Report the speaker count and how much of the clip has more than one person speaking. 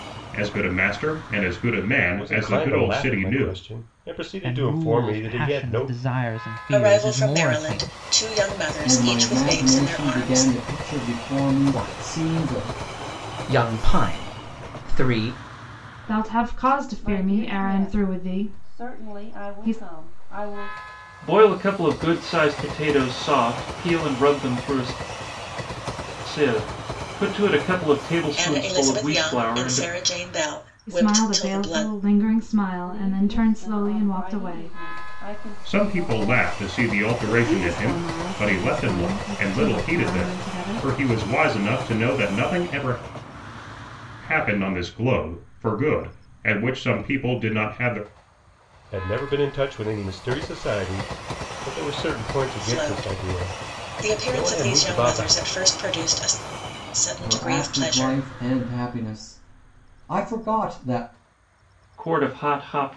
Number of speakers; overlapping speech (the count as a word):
nine, about 36%